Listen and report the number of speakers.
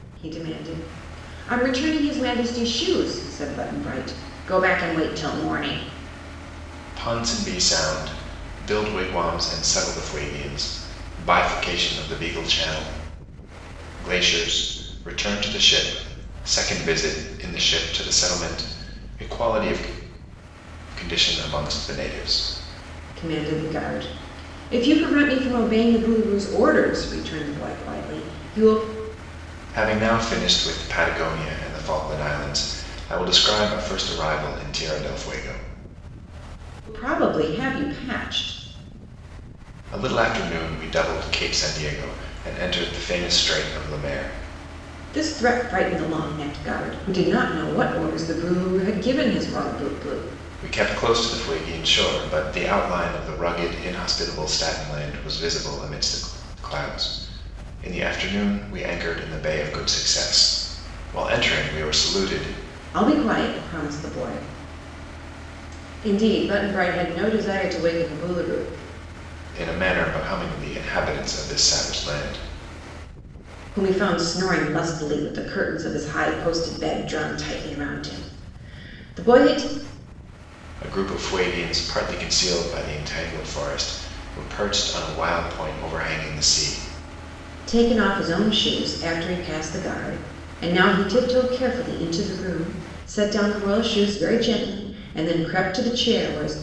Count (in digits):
2